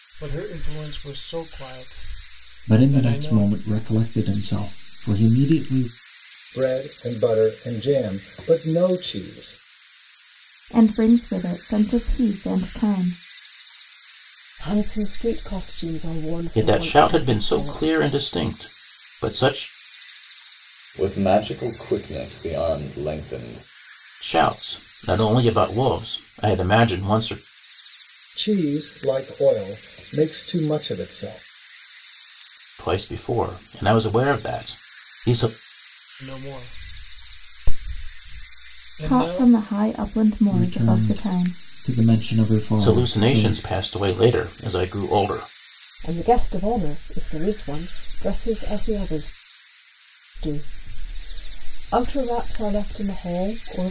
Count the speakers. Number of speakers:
seven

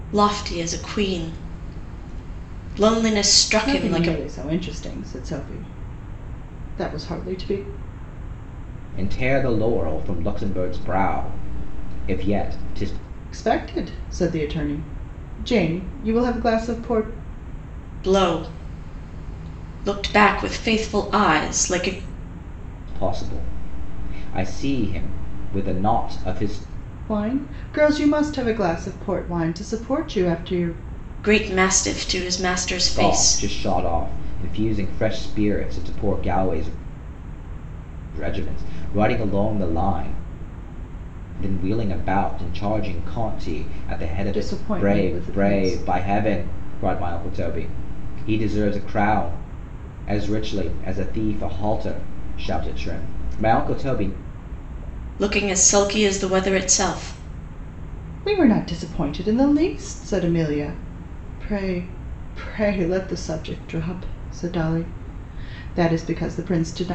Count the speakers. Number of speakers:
three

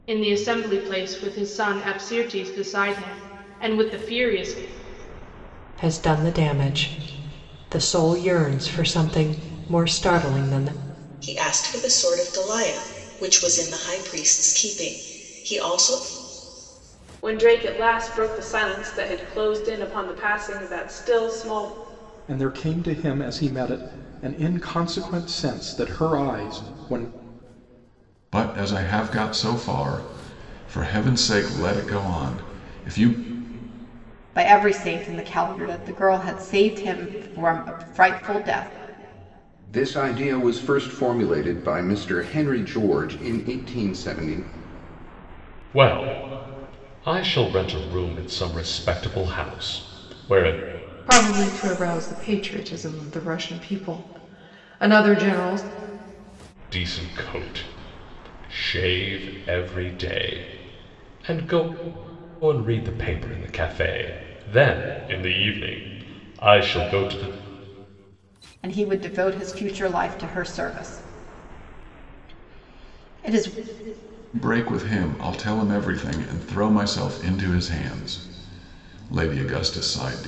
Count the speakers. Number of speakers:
ten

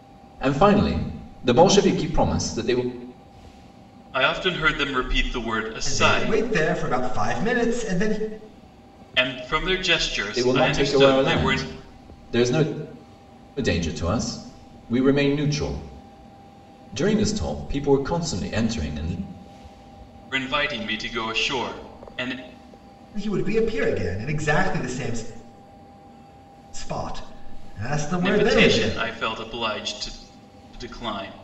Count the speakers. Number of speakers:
three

